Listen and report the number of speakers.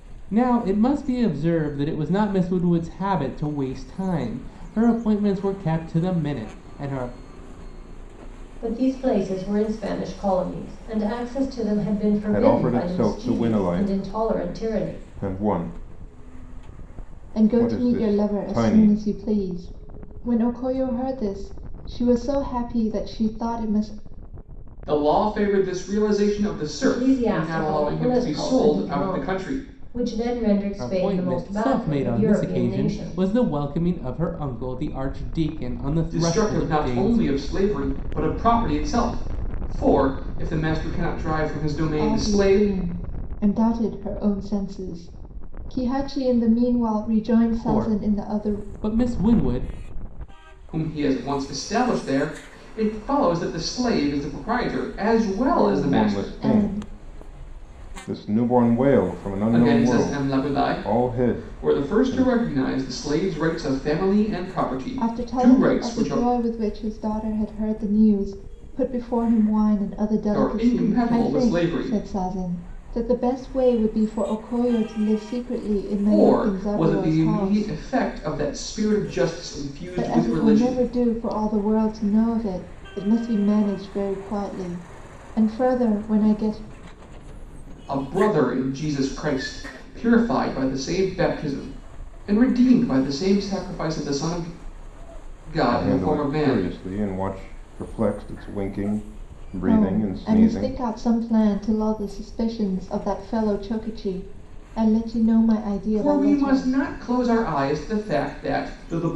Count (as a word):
five